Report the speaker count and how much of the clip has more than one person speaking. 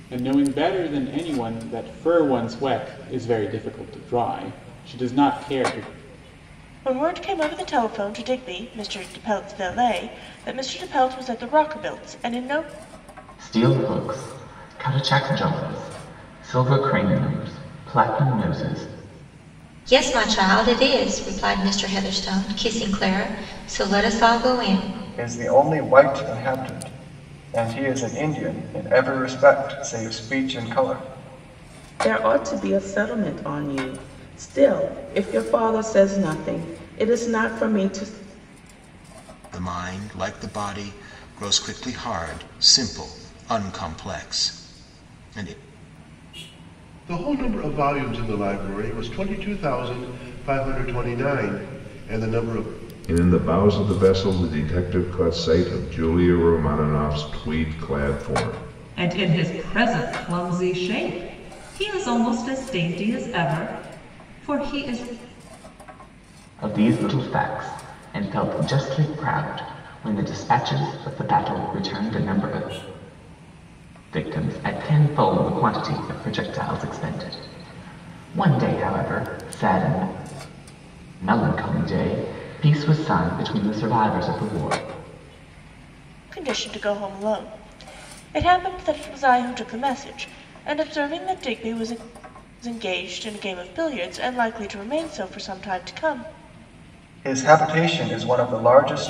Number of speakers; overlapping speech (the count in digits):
10, no overlap